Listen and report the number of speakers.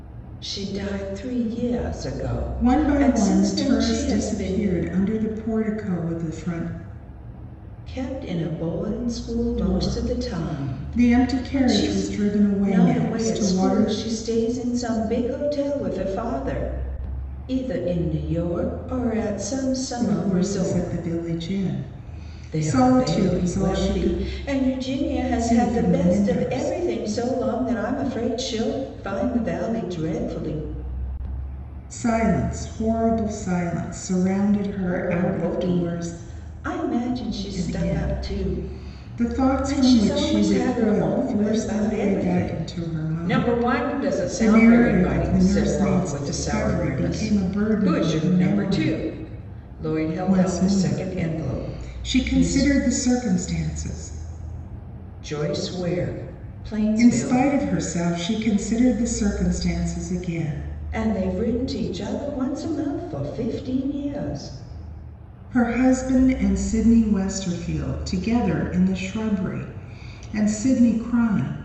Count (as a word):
two